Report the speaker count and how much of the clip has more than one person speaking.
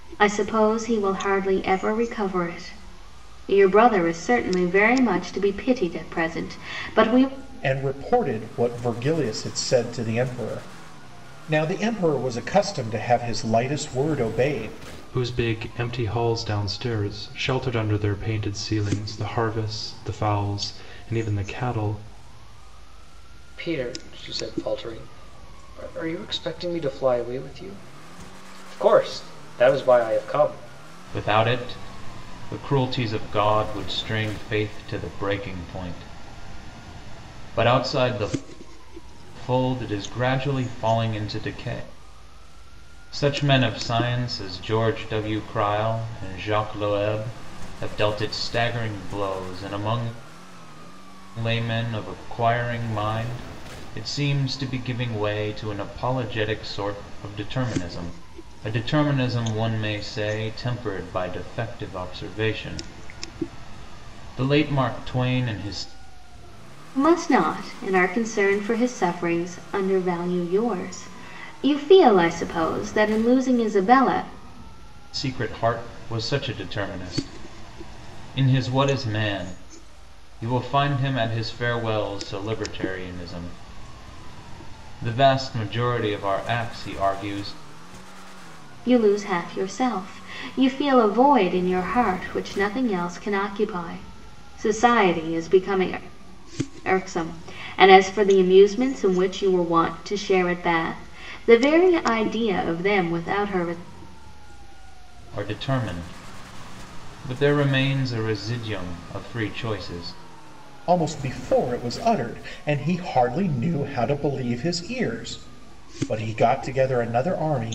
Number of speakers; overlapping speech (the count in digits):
5, no overlap